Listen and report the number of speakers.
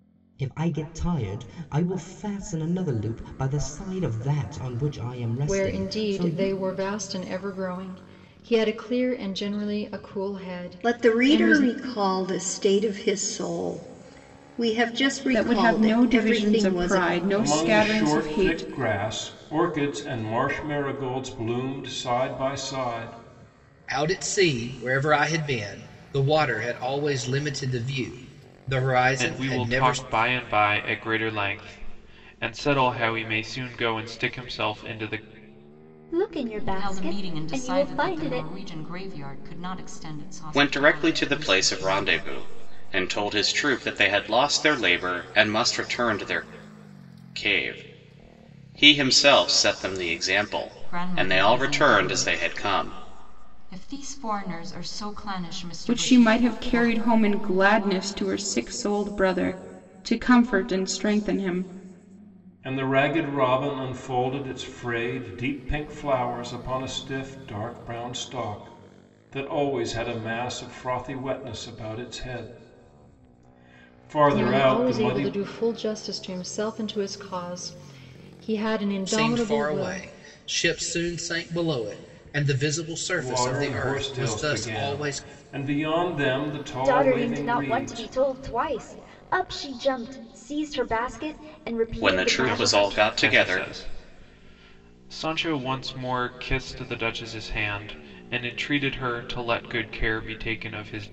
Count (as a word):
ten